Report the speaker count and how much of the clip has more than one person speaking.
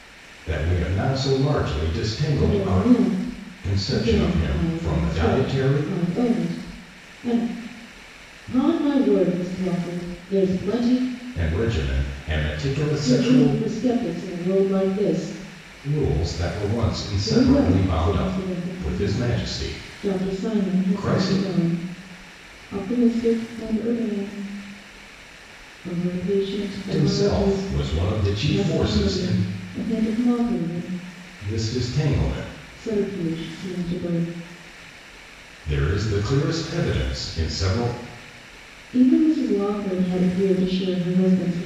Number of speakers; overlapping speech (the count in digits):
2, about 20%